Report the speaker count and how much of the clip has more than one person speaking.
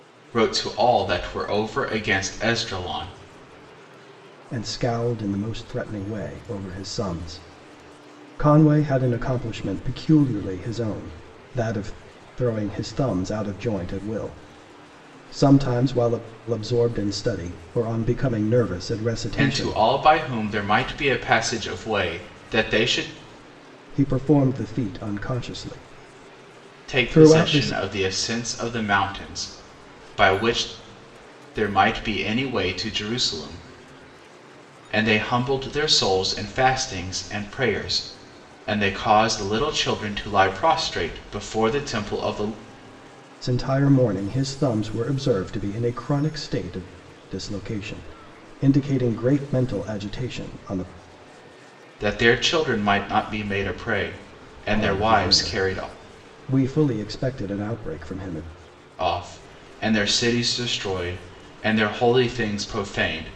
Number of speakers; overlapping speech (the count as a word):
two, about 4%